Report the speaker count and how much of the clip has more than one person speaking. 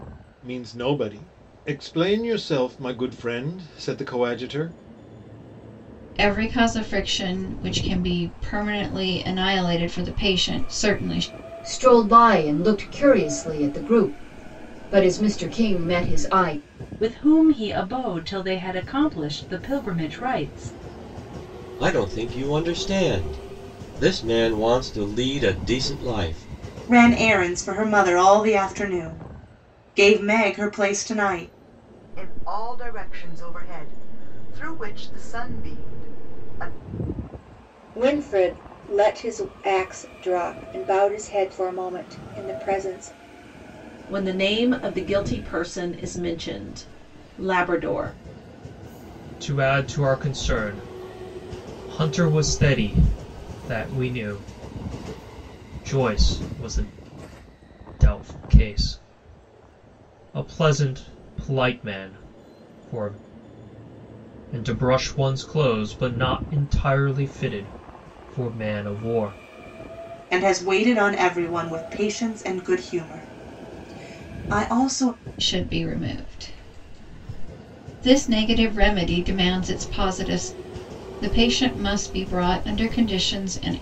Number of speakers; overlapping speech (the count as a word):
ten, no overlap